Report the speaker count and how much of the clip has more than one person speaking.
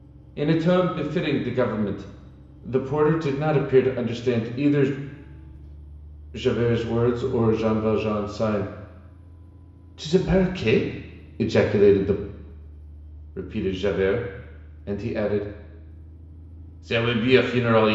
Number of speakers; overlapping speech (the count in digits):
1, no overlap